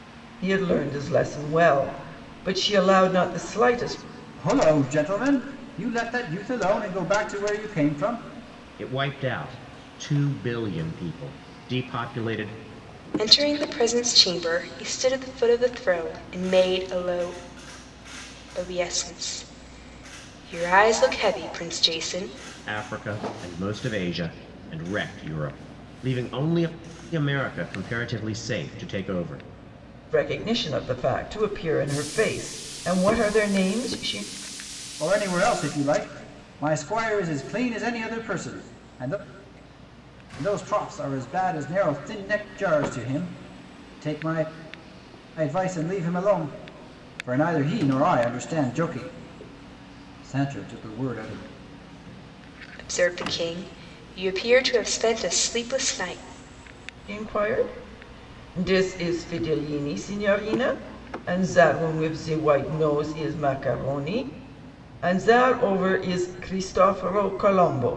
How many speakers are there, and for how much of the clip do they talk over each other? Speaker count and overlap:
4, no overlap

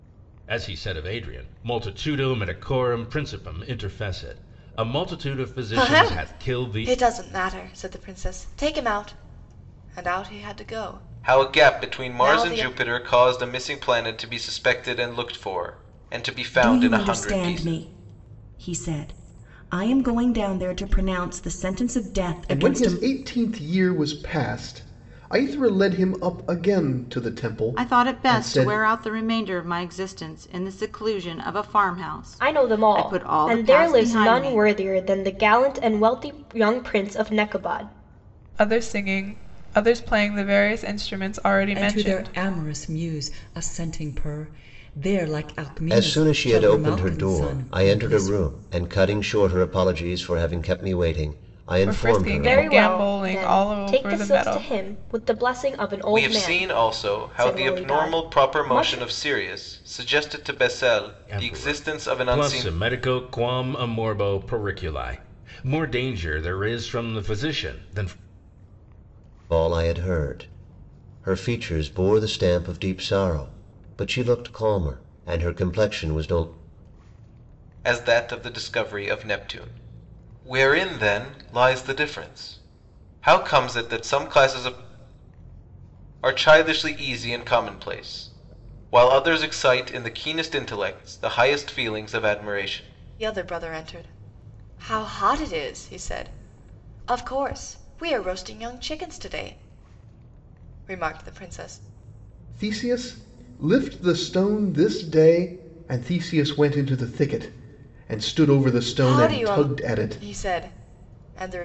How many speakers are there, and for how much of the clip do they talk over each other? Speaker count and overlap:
10, about 18%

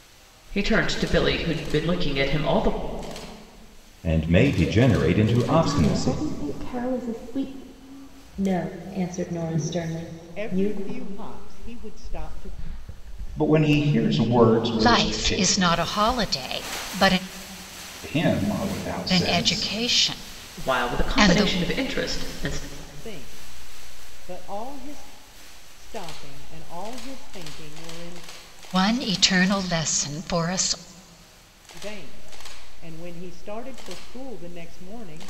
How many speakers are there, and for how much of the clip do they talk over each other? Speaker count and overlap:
7, about 10%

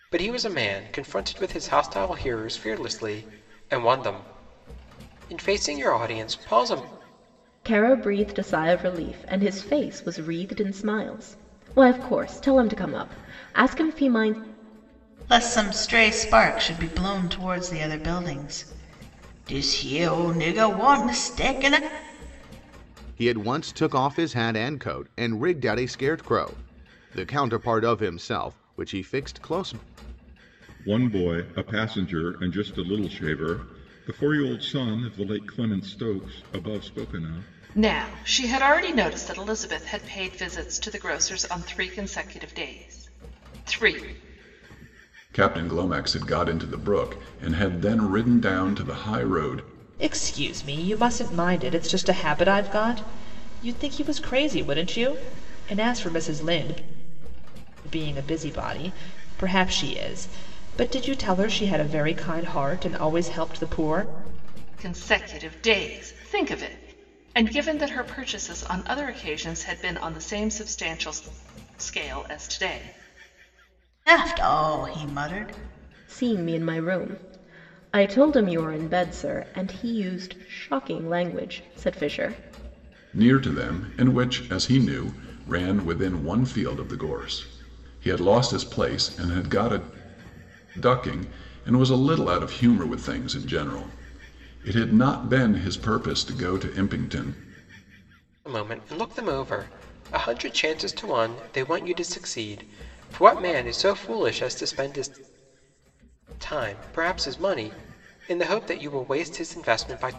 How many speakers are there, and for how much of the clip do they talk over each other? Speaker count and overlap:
8, no overlap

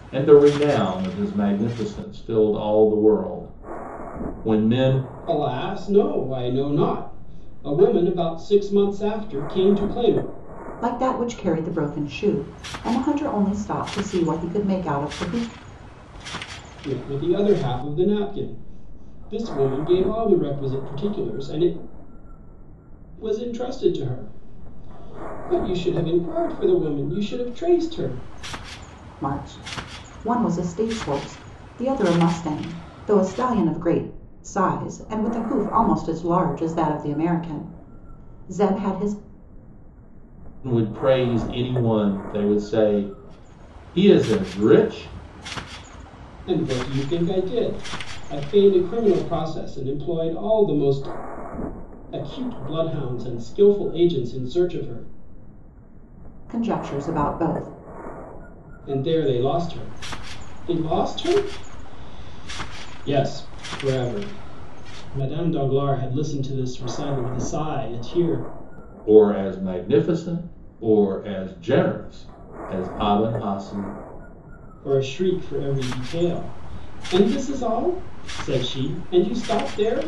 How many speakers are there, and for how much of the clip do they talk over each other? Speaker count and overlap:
3, no overlap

